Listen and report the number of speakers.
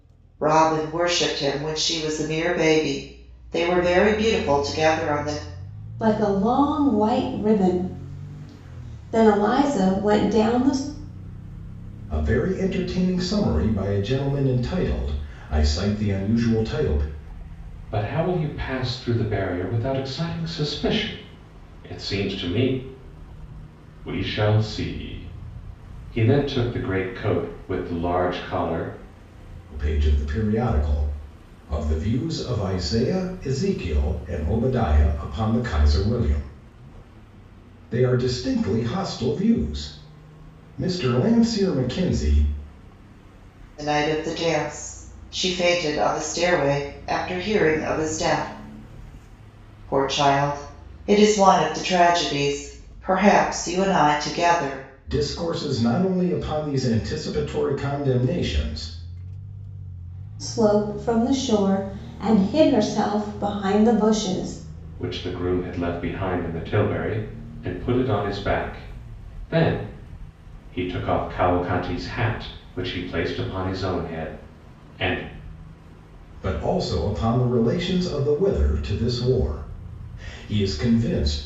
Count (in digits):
4